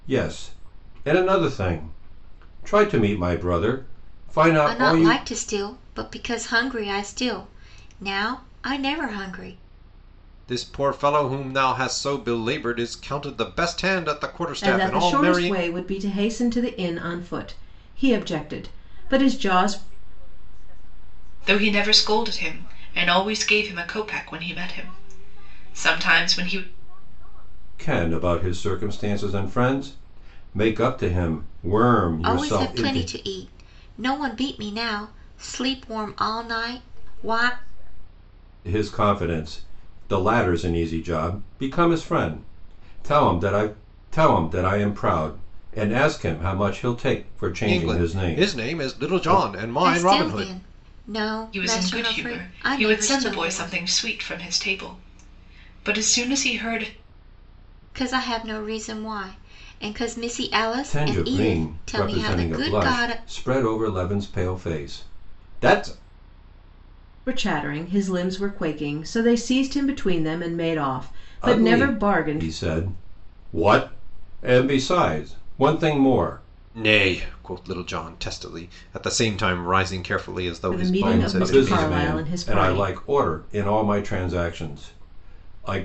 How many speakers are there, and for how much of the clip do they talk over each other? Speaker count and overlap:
6, about 23%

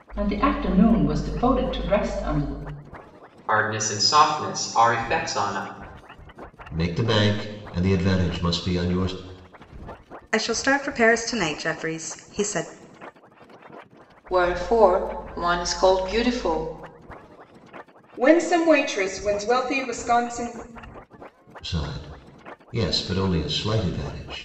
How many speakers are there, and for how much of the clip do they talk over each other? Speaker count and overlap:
6, no overlap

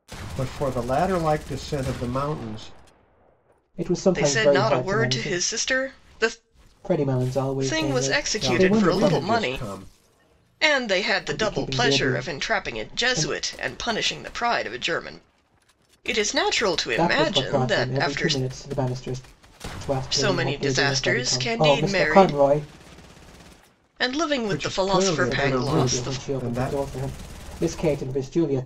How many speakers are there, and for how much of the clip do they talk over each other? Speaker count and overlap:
3, about 41%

